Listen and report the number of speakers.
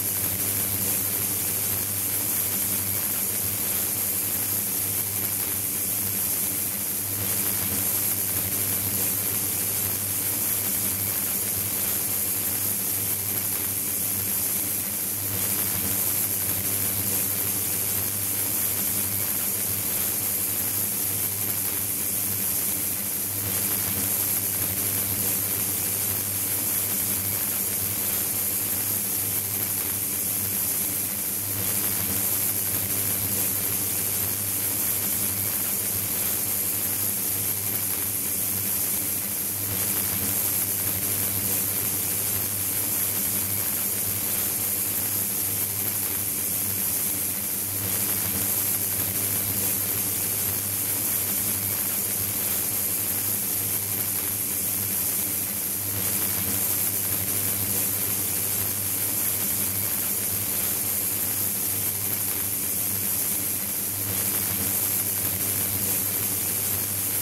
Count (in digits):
0